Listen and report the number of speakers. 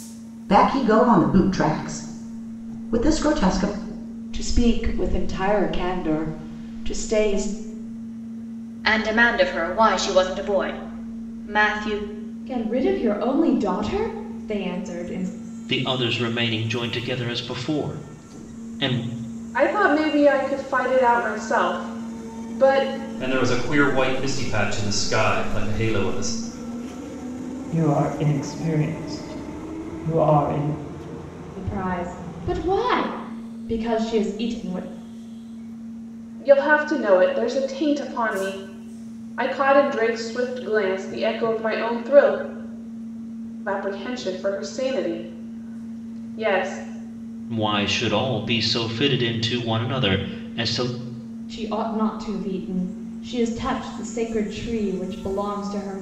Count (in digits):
8